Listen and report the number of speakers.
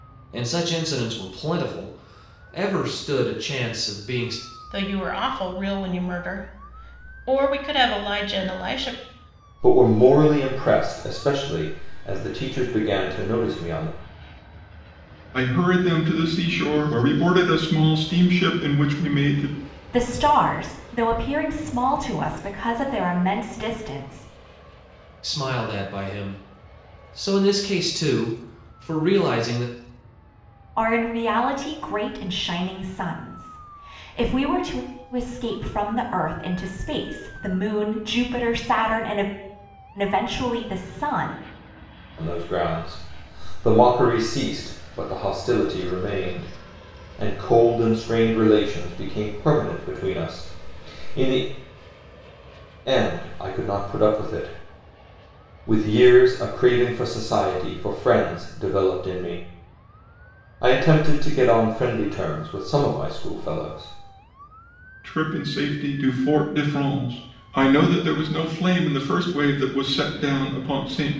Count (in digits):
5